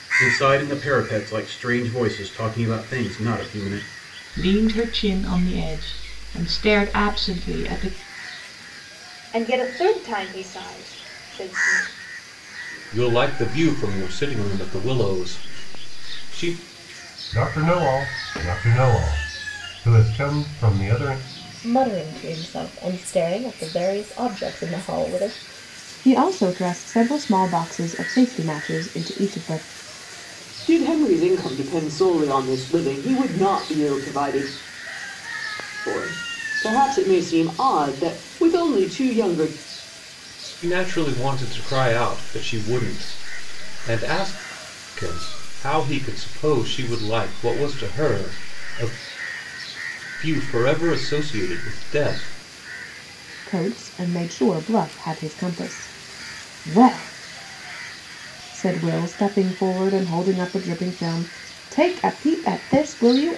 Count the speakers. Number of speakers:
eight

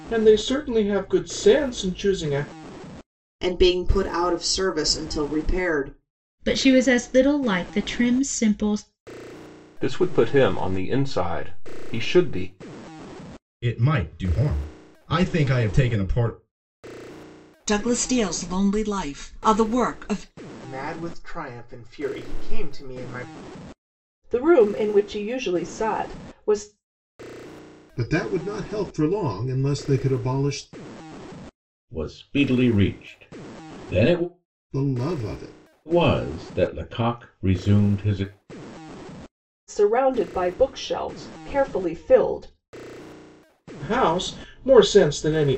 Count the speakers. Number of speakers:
ten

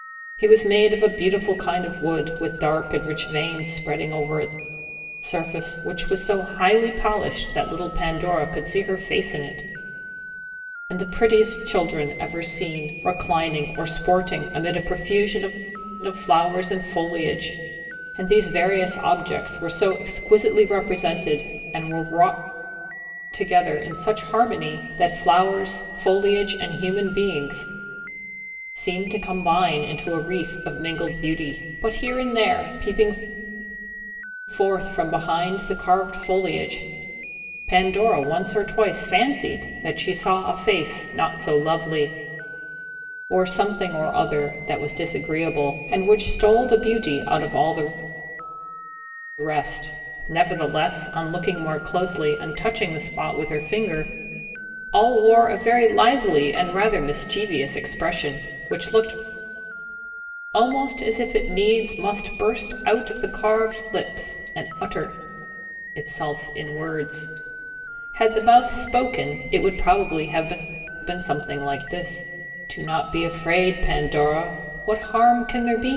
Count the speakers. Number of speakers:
one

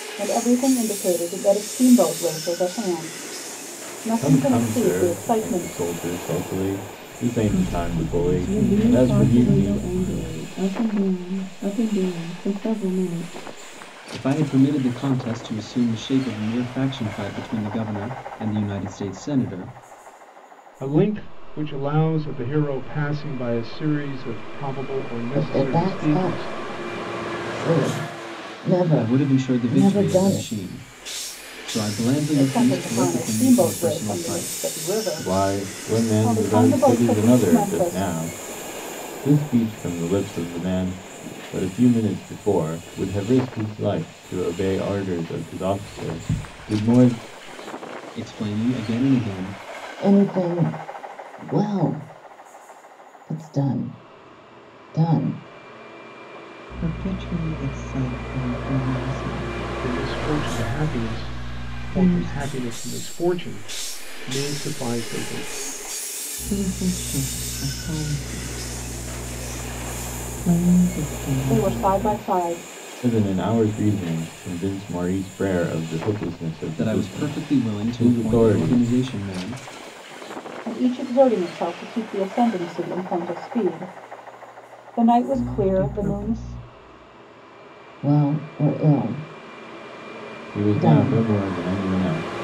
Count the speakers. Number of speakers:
seven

